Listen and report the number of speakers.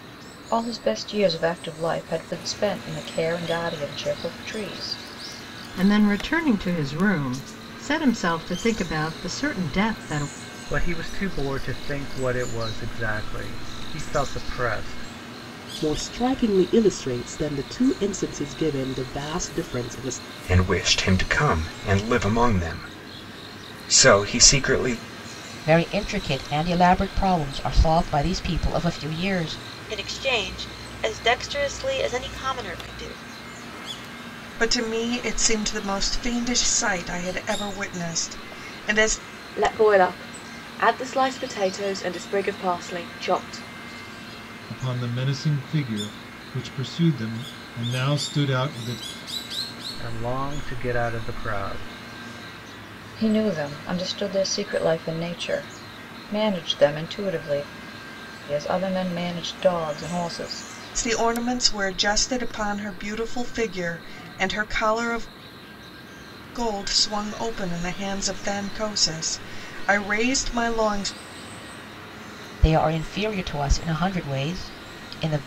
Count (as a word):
ten